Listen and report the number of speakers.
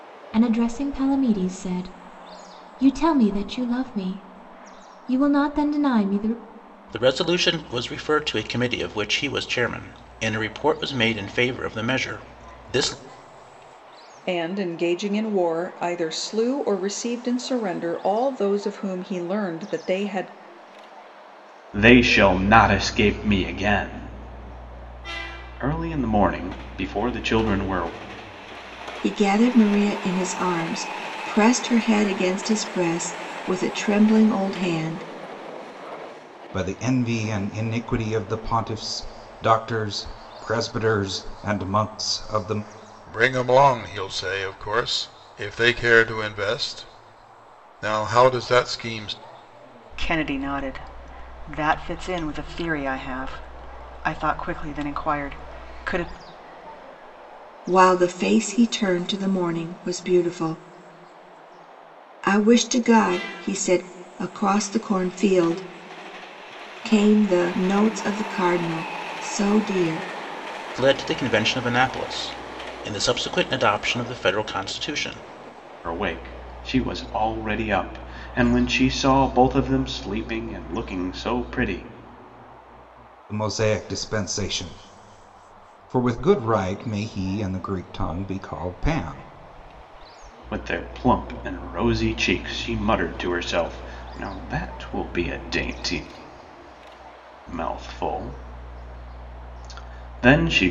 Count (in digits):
8